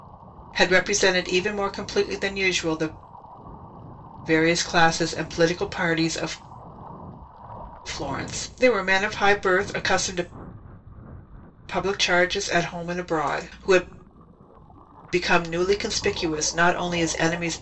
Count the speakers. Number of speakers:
one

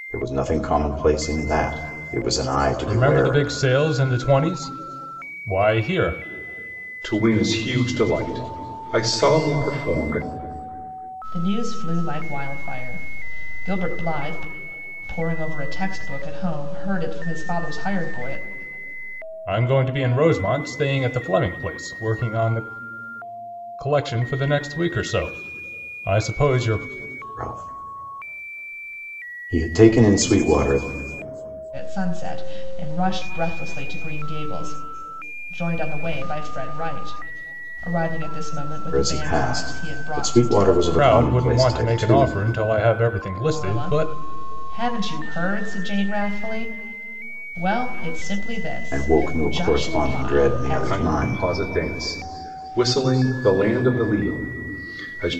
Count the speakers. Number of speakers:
four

